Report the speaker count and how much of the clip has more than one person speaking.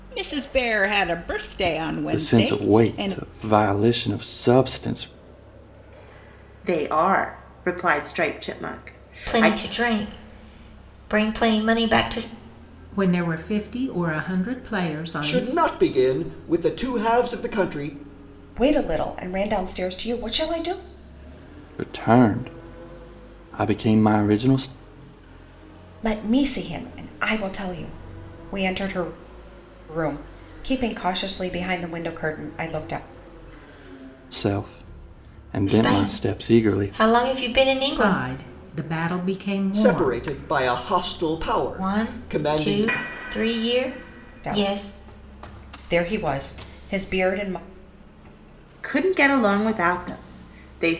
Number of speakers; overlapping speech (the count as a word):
seven, about 11%